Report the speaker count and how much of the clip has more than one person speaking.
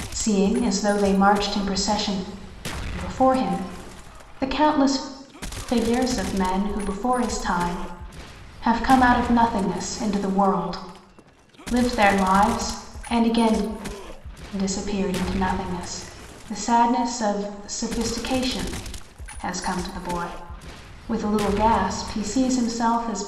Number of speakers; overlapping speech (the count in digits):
1, no overlap